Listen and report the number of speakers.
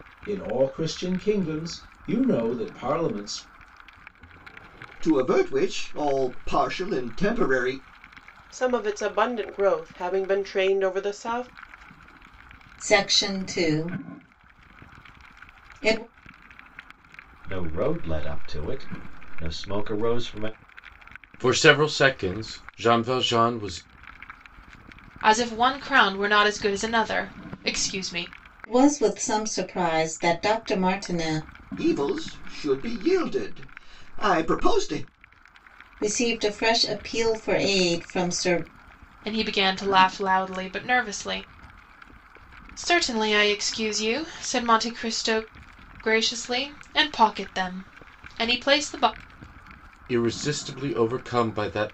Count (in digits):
7